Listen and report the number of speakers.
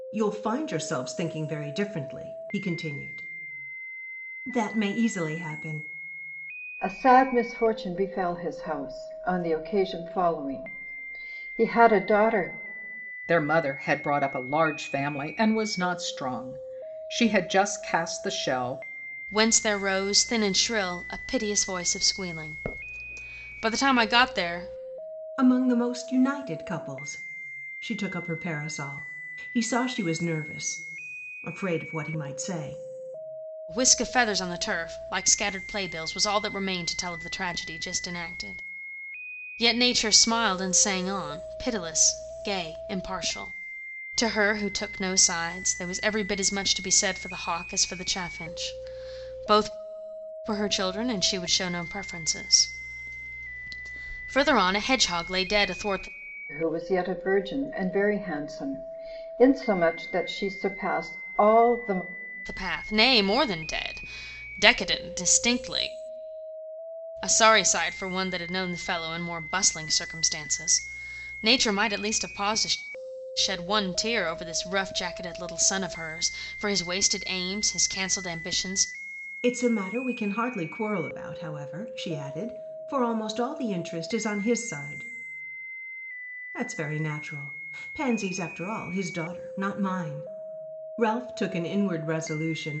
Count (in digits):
4